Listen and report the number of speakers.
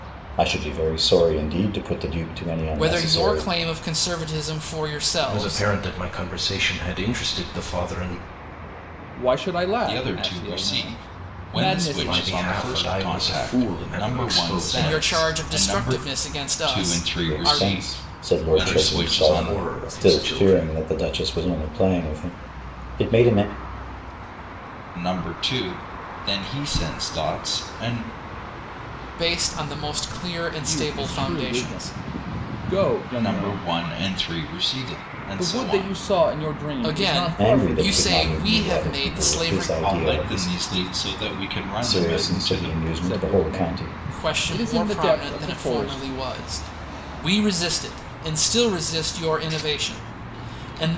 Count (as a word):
five